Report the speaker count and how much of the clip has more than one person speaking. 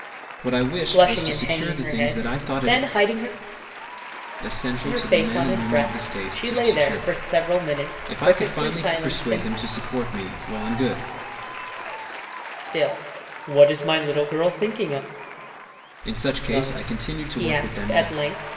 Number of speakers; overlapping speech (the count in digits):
2, about 45%